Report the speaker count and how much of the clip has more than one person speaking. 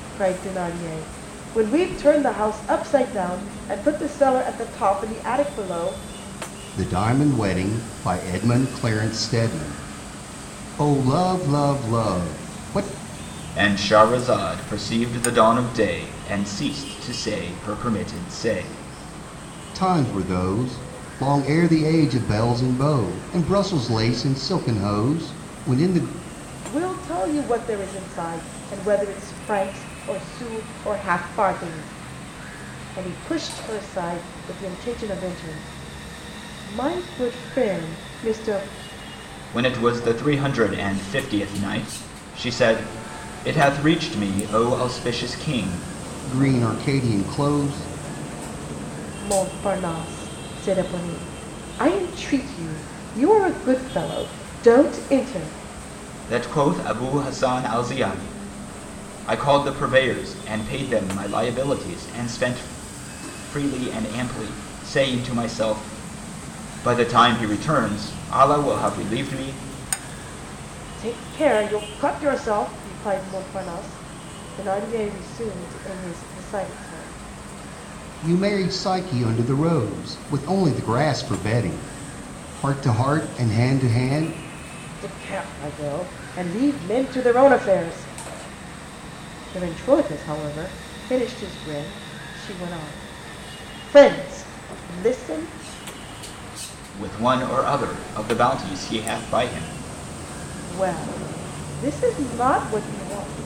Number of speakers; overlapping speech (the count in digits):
3, no overlap